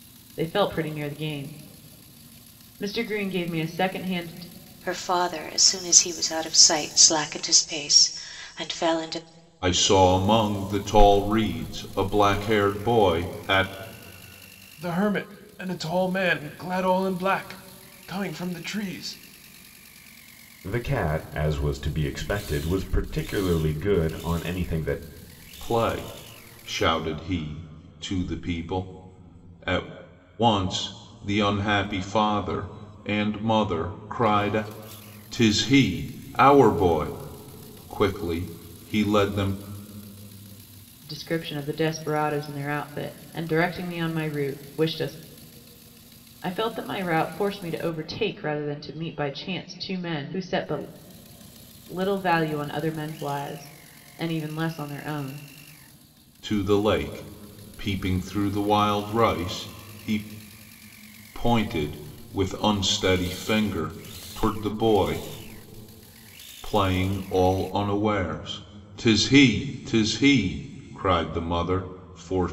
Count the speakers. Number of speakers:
5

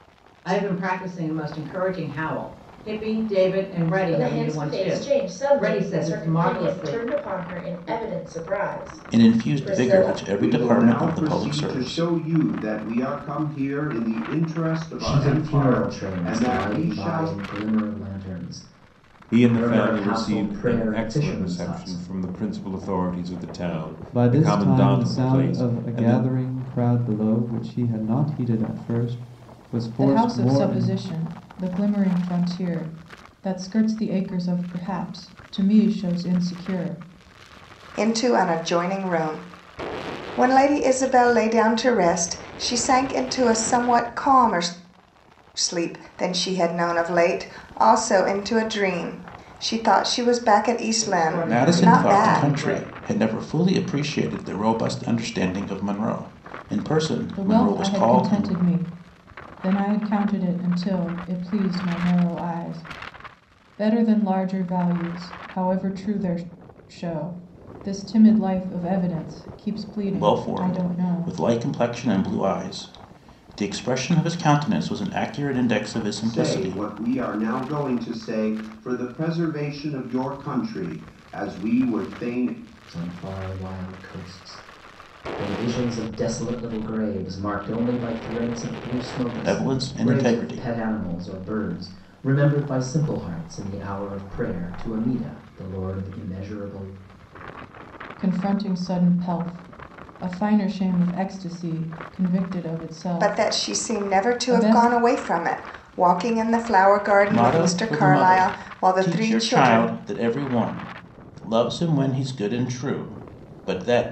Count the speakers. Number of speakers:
9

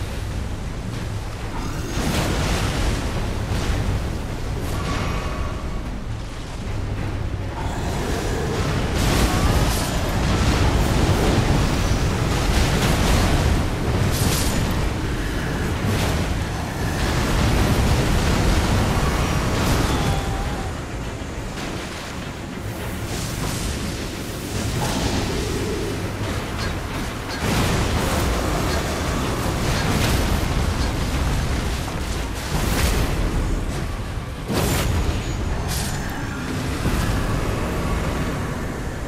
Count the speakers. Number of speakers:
0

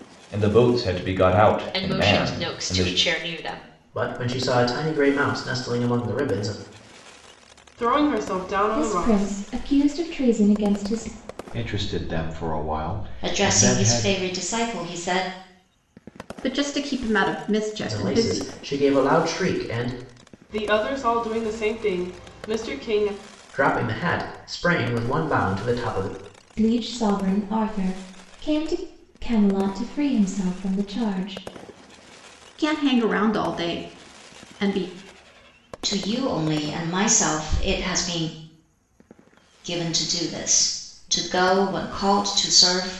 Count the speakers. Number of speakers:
8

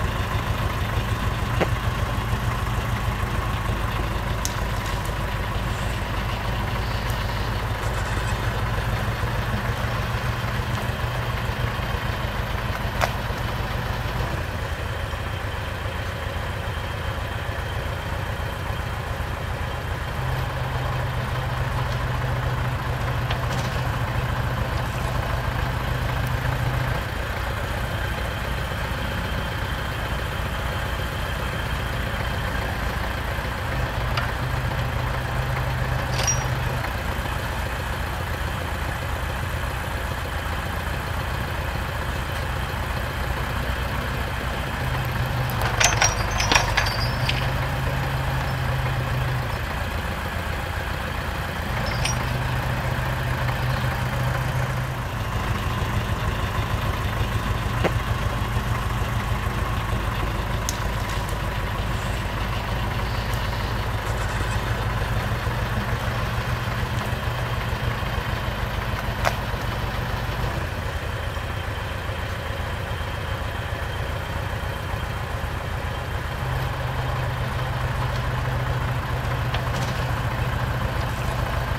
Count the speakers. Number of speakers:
0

